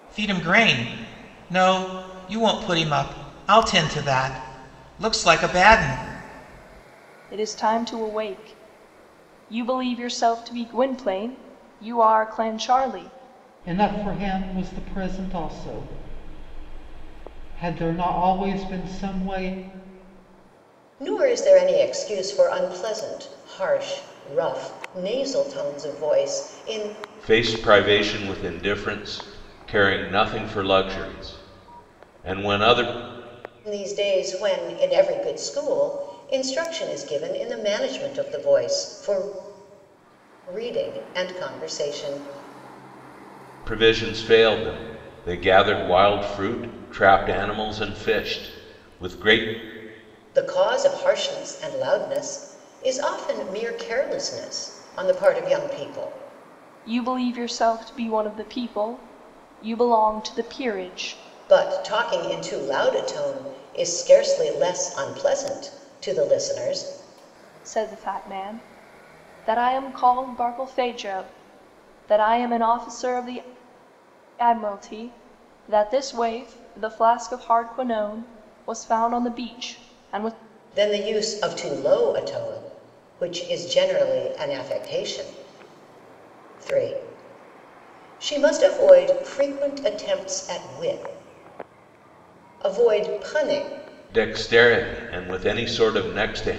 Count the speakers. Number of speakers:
5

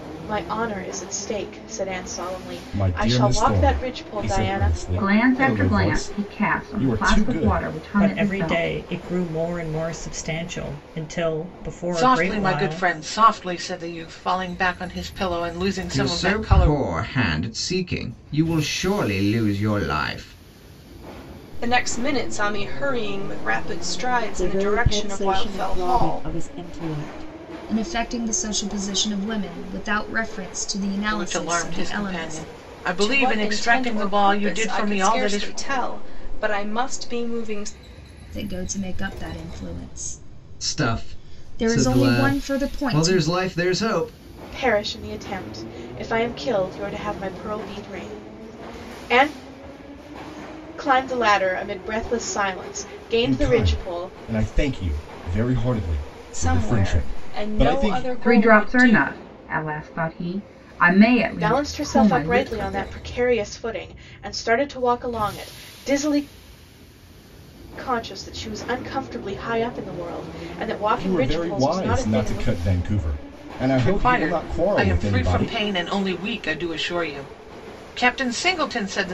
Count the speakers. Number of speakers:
9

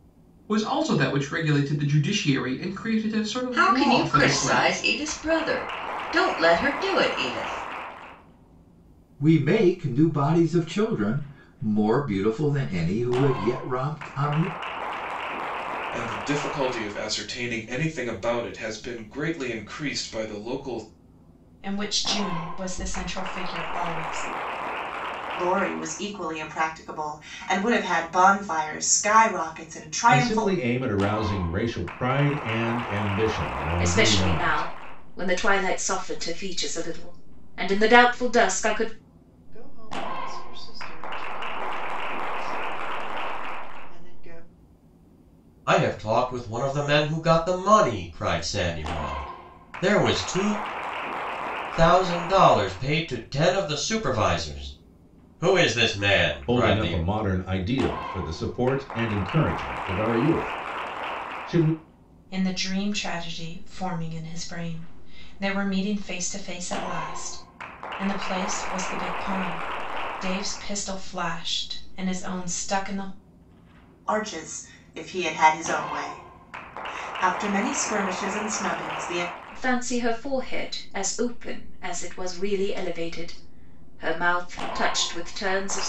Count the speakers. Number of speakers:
10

